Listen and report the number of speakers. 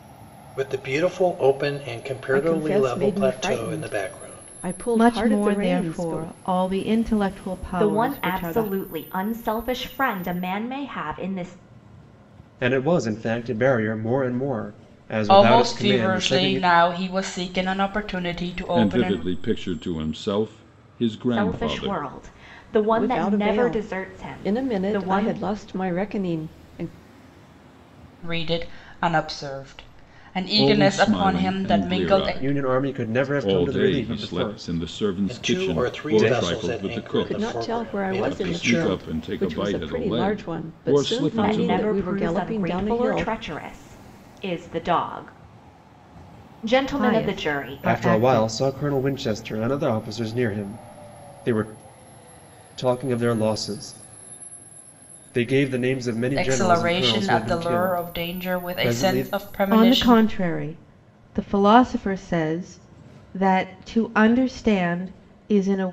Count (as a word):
seven